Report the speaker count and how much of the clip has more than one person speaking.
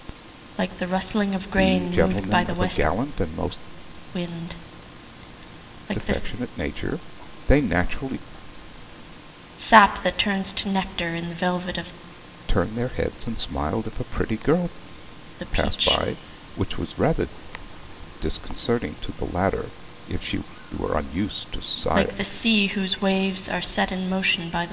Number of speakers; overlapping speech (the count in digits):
2, about 11%